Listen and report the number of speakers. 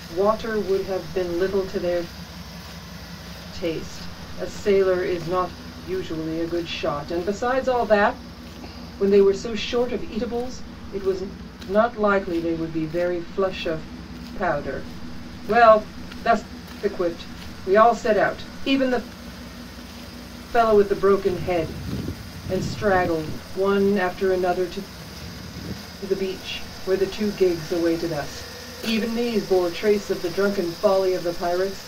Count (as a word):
one